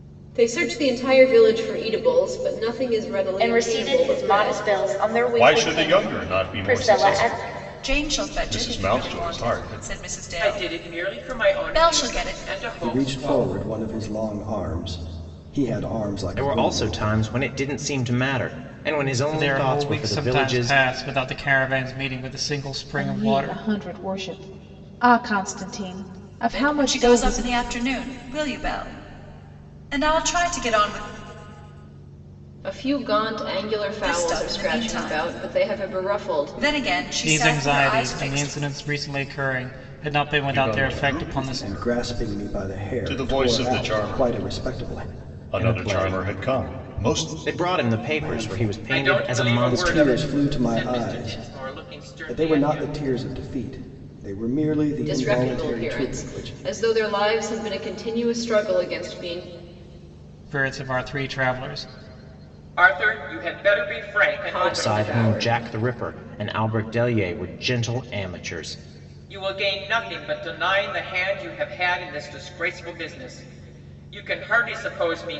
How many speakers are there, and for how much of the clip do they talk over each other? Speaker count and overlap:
9, about 38%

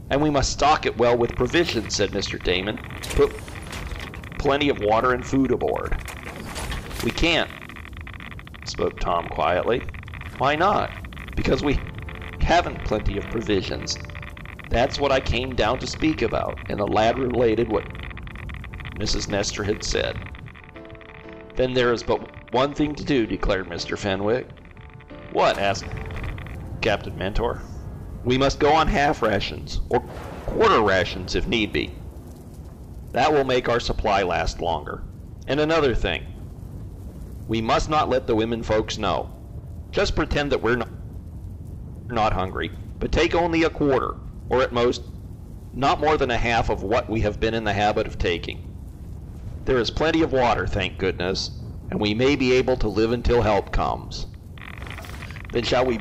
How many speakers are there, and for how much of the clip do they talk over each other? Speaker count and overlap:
1, no overlap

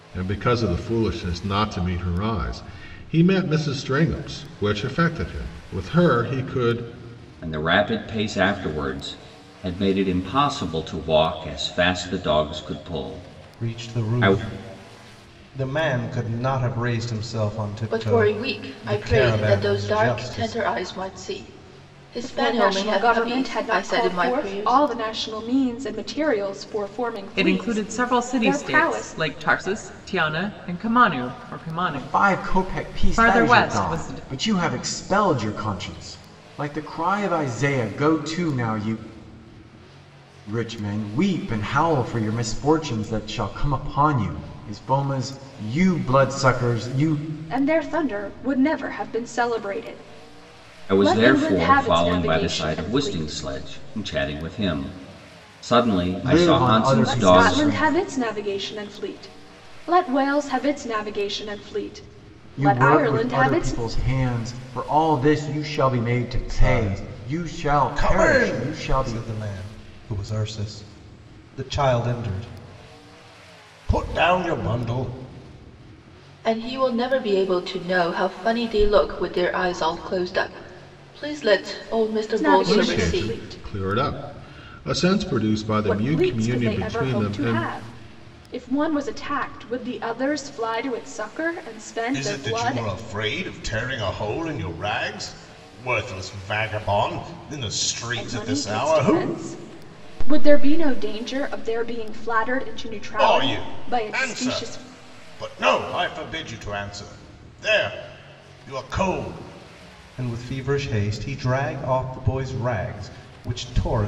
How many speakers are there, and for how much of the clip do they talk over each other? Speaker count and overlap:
7, about 22%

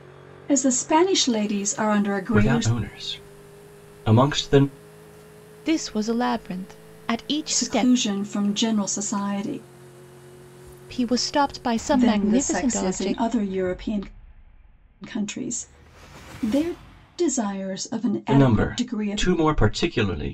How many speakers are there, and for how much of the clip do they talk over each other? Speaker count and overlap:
3, about 16%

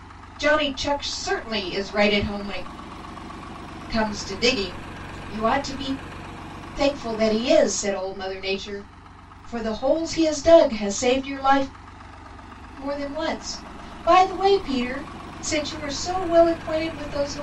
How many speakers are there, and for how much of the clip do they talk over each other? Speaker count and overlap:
1, no overlap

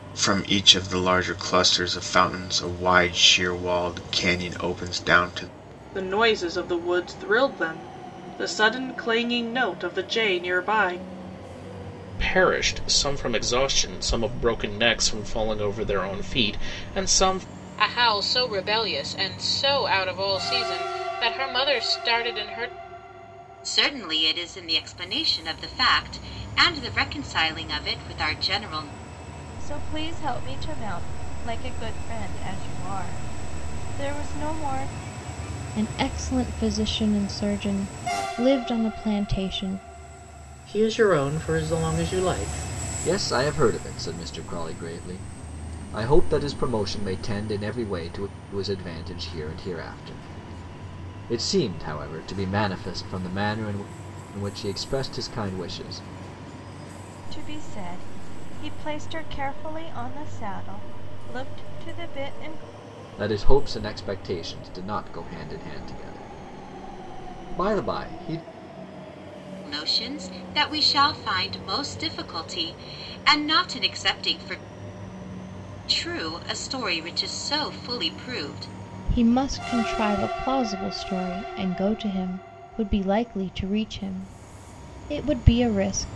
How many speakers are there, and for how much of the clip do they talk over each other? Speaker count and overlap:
9, no overlap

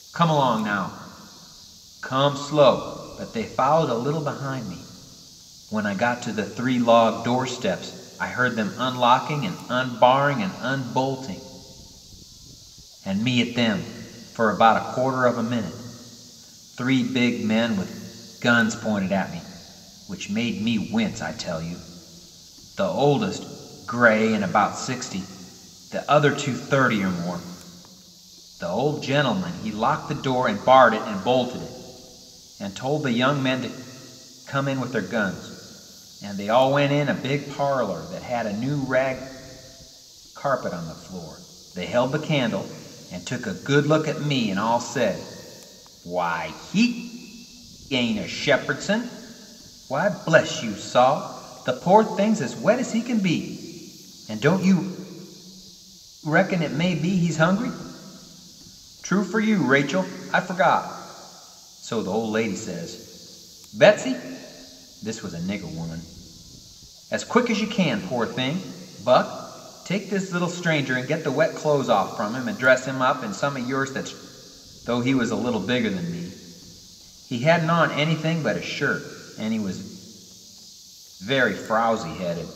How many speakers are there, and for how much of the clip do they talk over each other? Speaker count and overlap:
1, no overlap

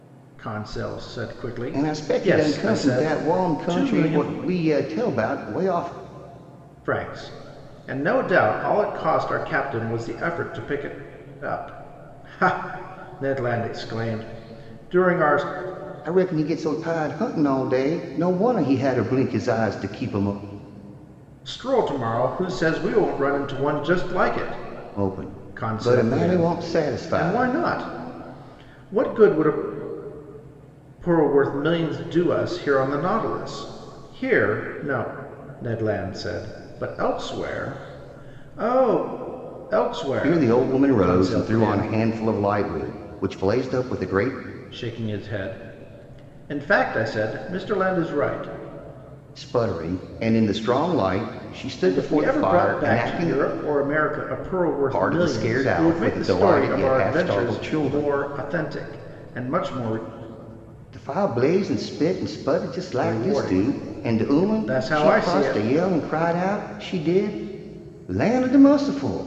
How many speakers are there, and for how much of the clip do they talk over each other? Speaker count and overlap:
2, about 20%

